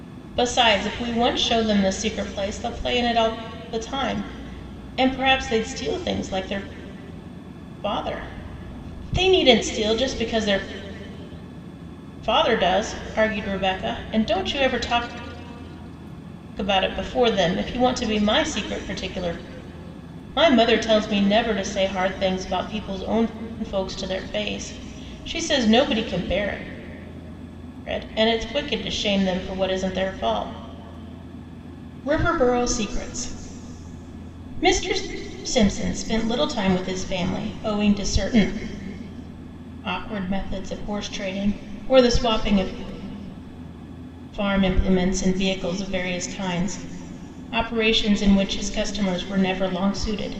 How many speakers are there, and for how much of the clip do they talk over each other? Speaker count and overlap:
one, no overlap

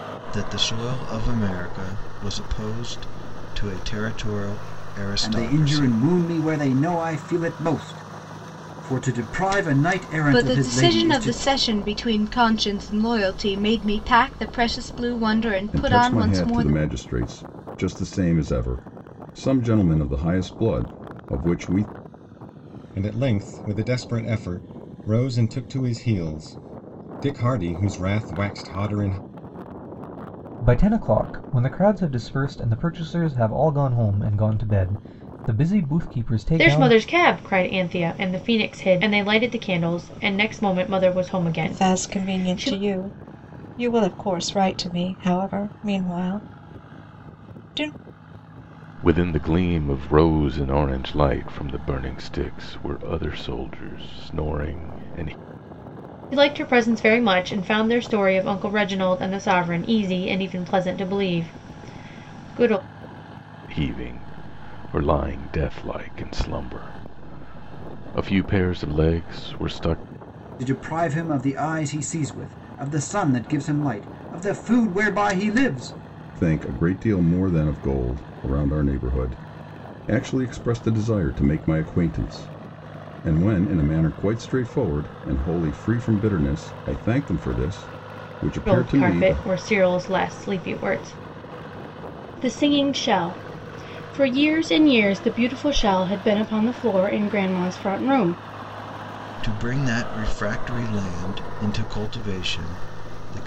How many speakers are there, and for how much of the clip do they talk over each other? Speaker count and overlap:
nine, about 5%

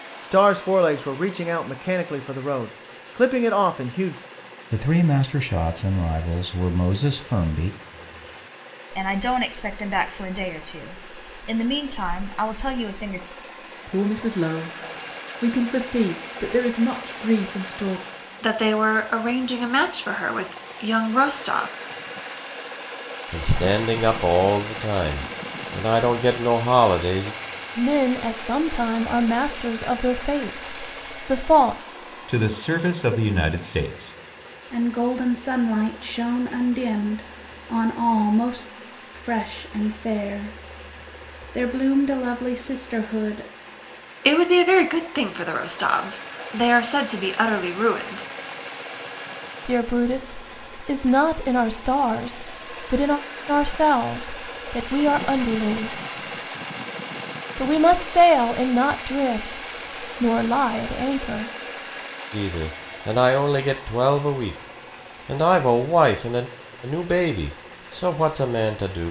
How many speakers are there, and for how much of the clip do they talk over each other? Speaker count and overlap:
nine, no overlap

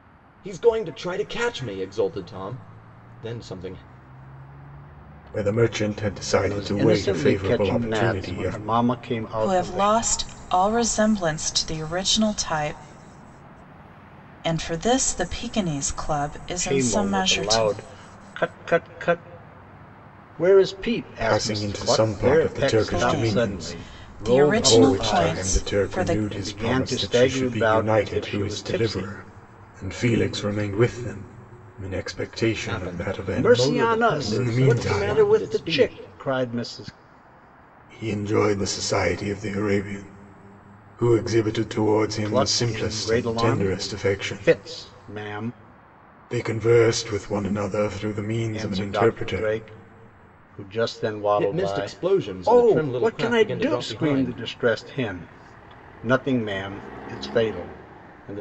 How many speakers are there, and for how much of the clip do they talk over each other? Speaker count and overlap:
four, about 37%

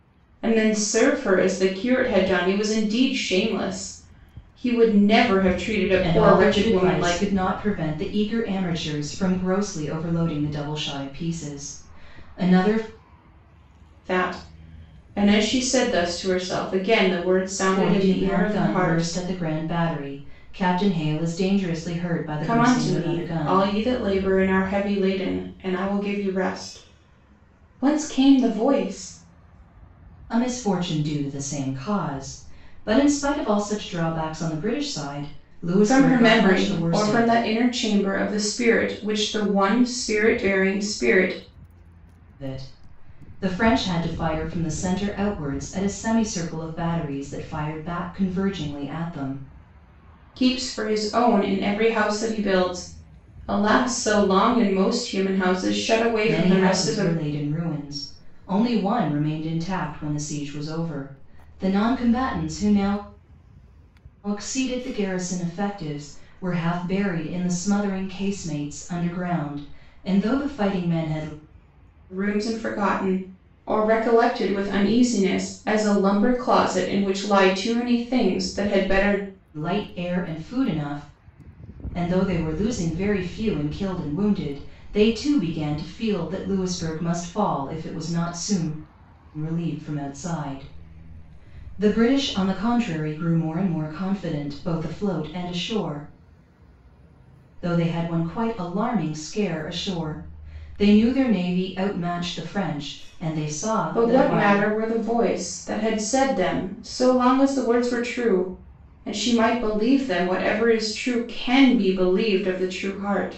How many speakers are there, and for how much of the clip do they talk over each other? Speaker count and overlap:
two, about 6%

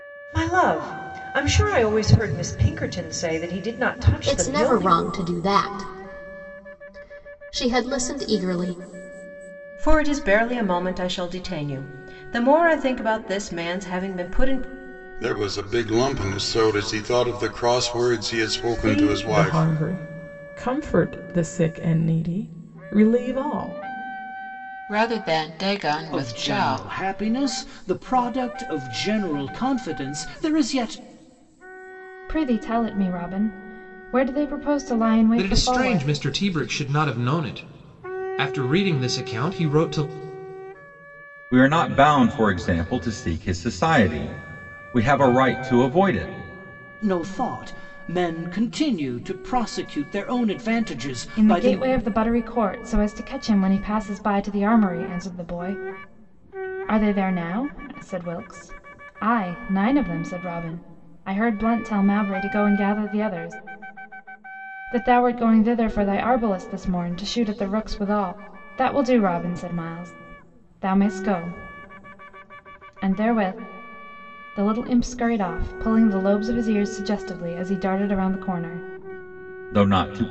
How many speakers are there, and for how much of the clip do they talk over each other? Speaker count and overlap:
ten, about 5%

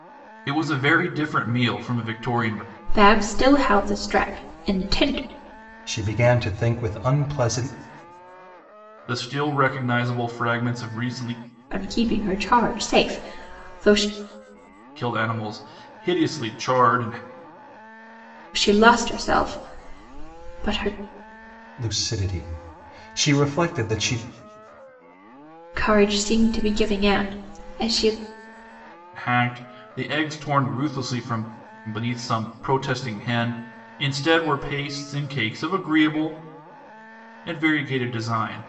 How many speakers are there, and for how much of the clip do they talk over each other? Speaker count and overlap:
three, no overlap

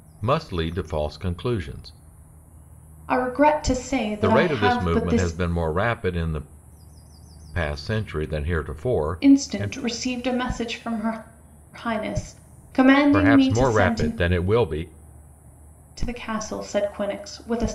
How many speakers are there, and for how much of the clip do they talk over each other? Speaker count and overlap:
two, about 17%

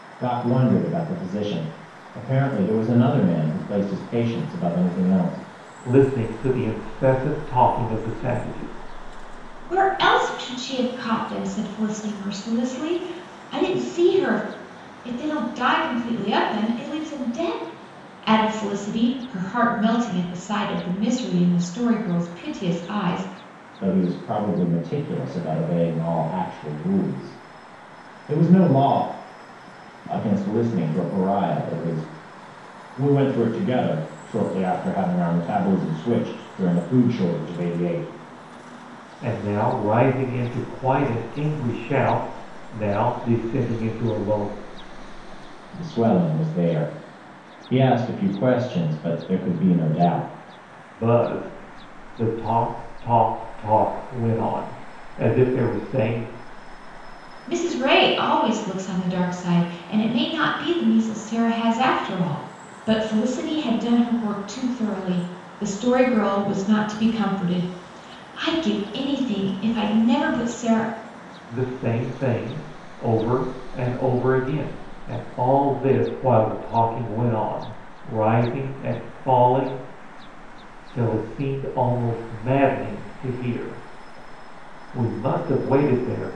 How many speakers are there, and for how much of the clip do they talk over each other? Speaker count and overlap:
three, no overlap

